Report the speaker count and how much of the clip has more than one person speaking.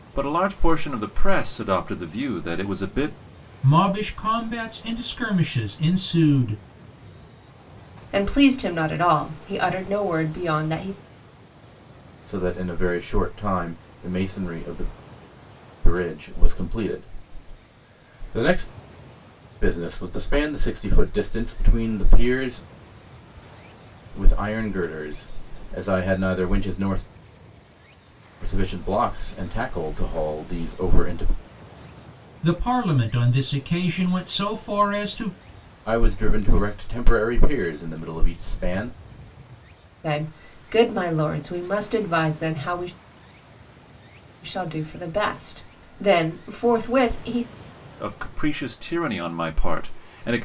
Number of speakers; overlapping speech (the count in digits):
4, no overlap